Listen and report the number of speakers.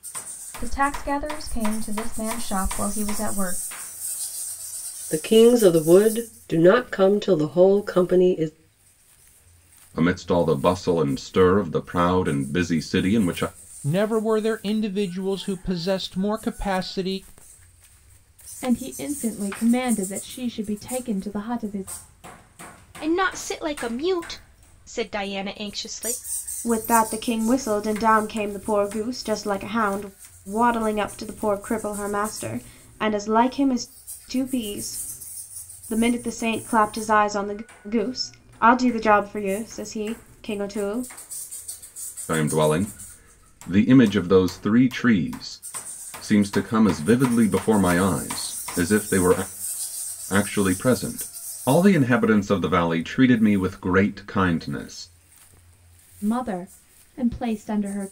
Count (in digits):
7